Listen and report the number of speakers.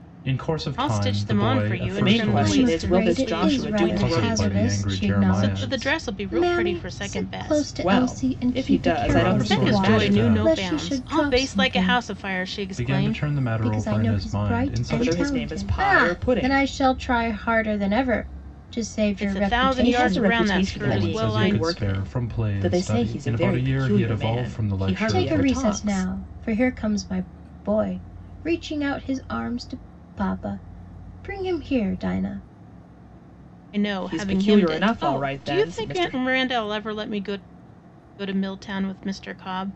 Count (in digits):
4